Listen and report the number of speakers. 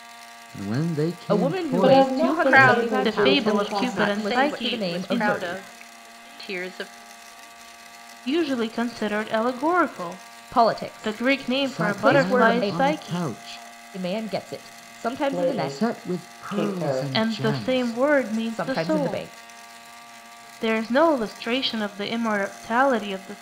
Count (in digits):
5